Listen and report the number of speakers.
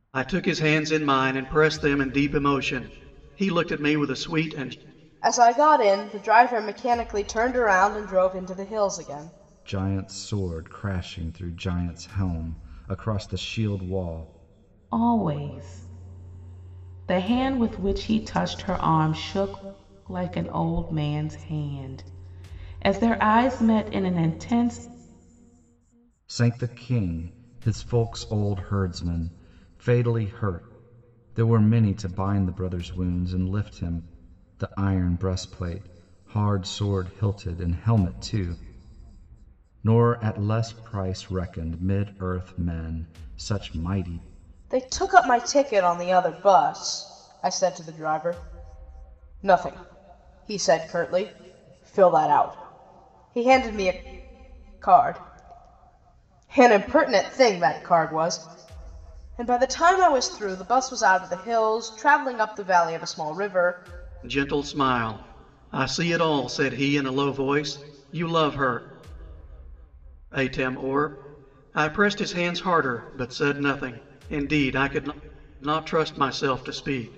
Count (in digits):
4